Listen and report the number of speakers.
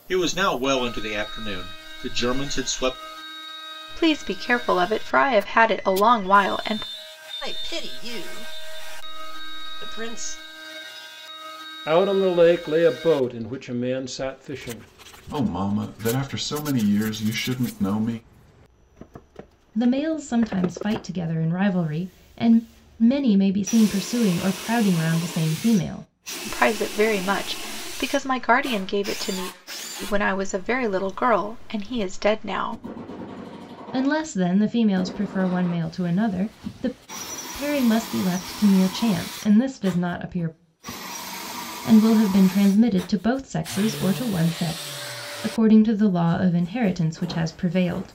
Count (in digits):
6